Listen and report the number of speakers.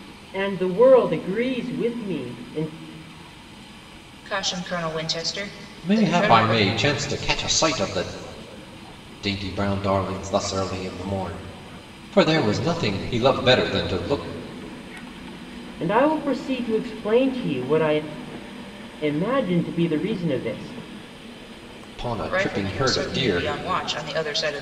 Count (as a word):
three